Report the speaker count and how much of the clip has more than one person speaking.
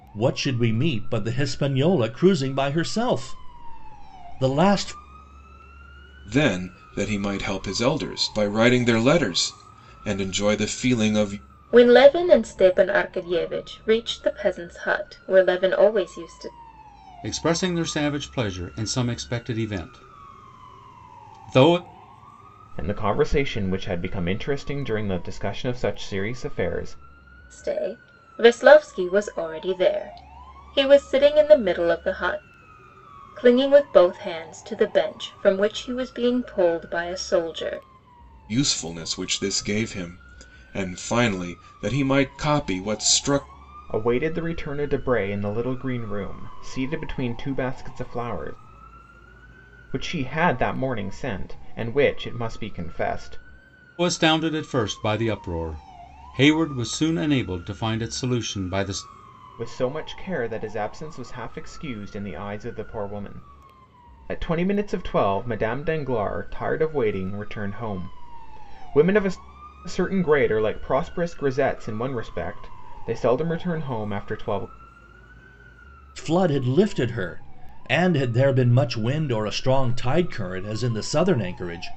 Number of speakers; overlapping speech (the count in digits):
5, no overlap